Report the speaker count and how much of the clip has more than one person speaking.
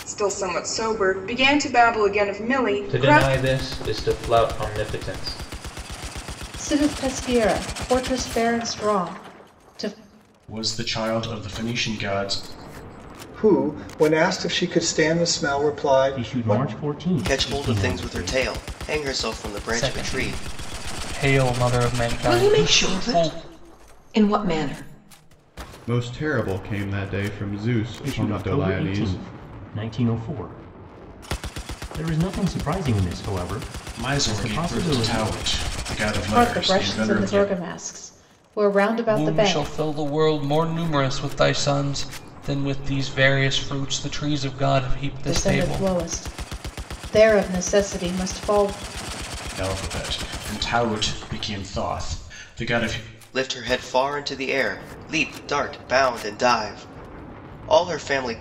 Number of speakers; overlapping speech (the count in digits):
10, about 16%